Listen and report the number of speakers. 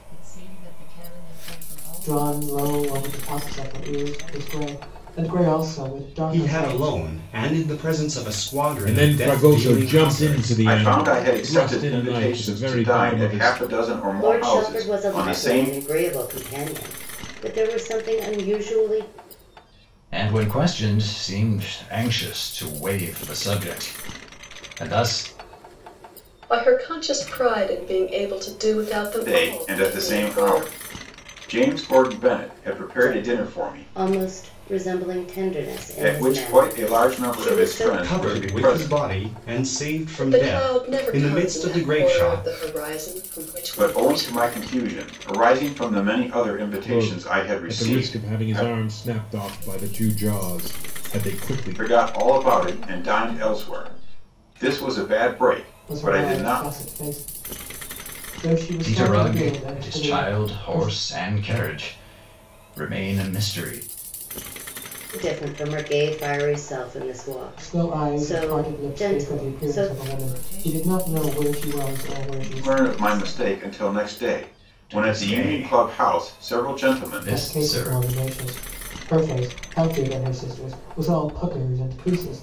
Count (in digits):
8